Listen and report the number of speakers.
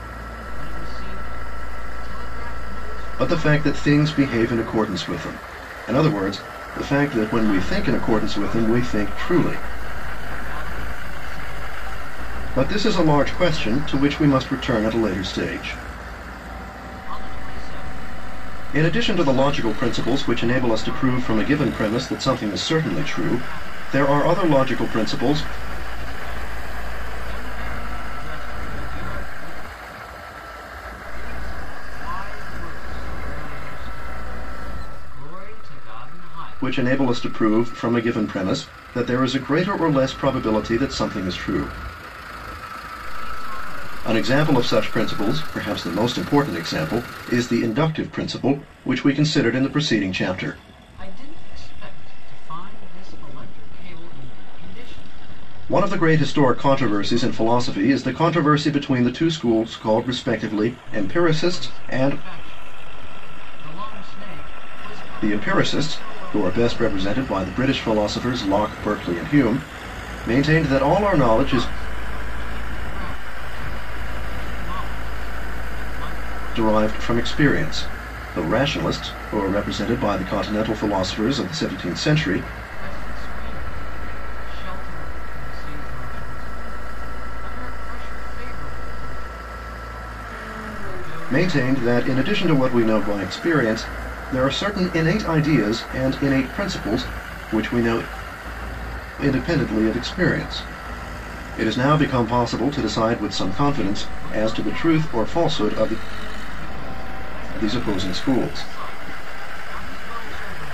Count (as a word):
two